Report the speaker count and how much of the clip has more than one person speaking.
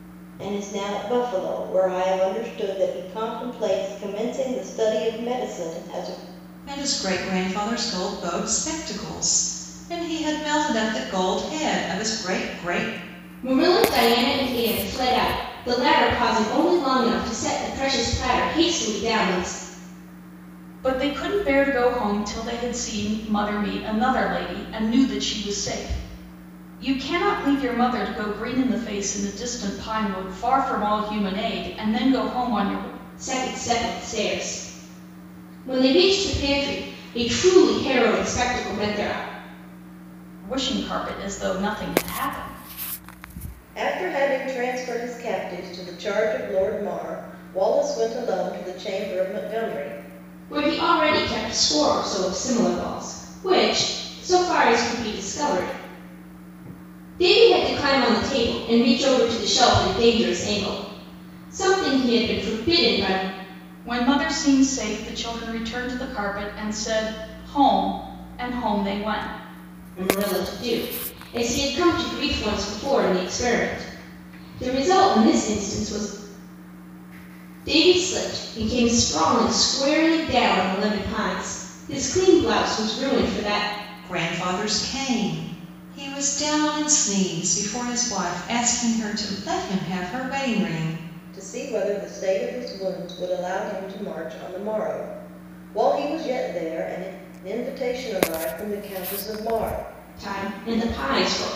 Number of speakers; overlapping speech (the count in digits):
4, no overlap